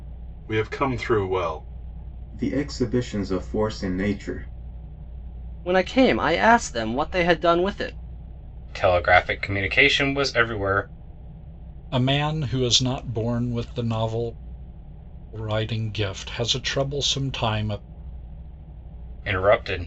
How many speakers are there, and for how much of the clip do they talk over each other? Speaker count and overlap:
five, no overlap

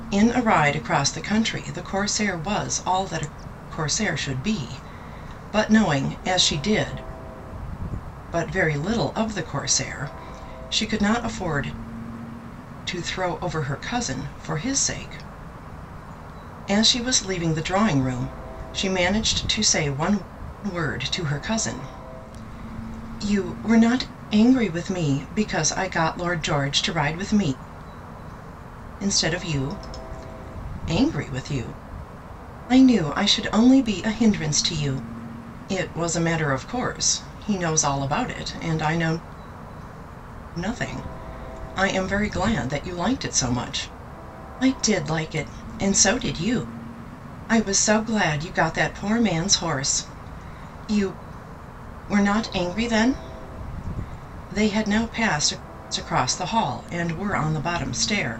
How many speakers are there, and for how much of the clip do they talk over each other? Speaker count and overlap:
one, no overlap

